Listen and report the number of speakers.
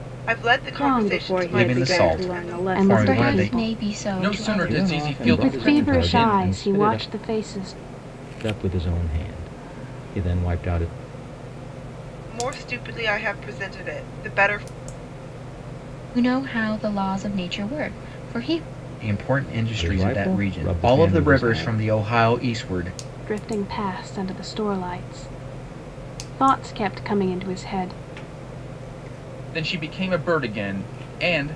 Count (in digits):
7